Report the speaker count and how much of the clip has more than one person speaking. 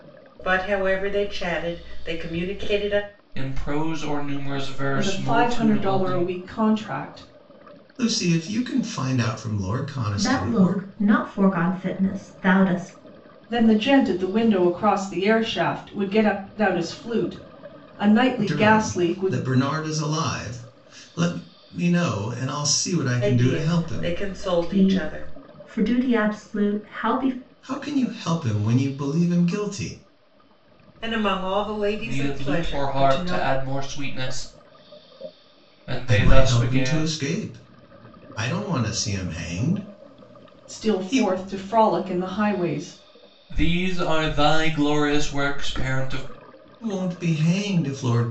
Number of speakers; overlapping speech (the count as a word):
five, about 16%